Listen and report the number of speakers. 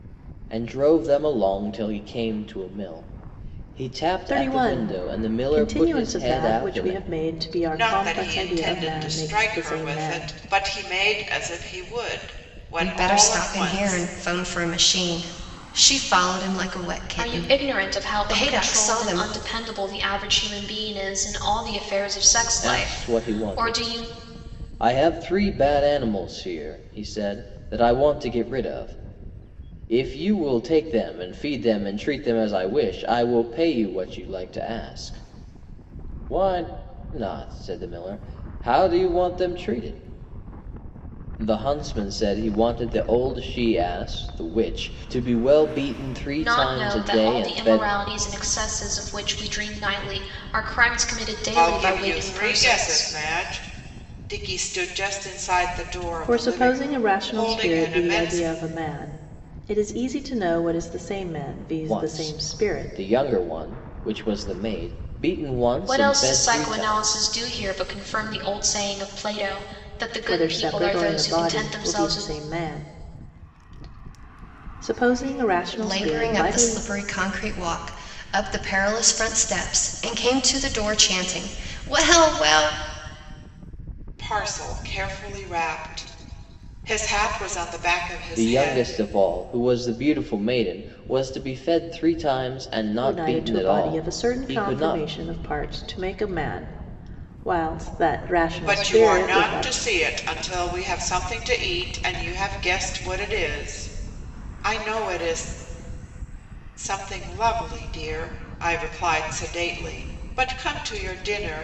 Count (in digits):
5